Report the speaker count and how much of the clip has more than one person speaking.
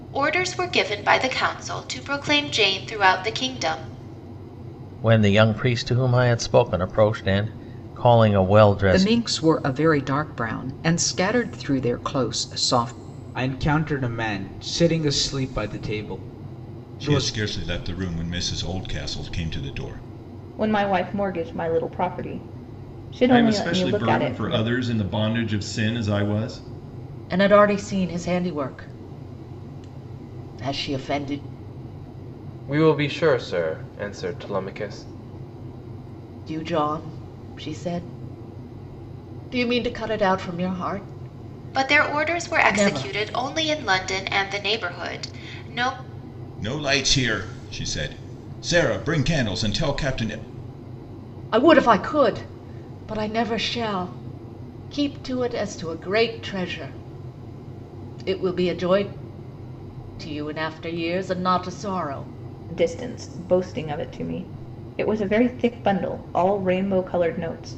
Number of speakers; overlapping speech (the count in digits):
9, about 5%